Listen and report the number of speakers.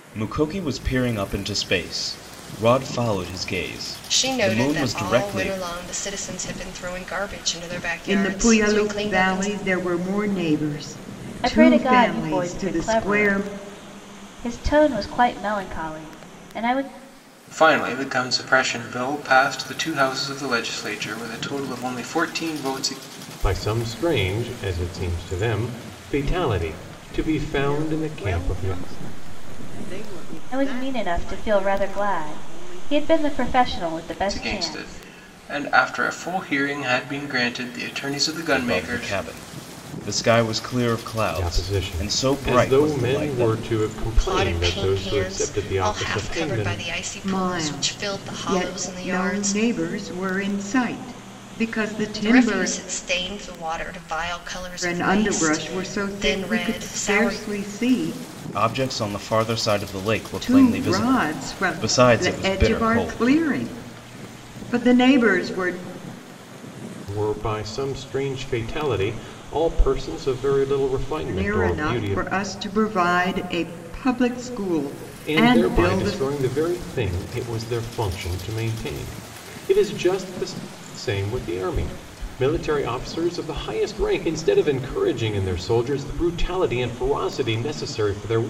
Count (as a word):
seven